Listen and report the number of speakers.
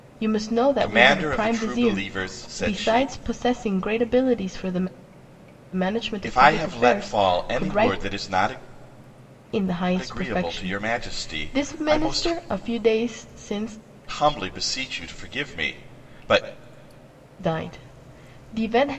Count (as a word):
two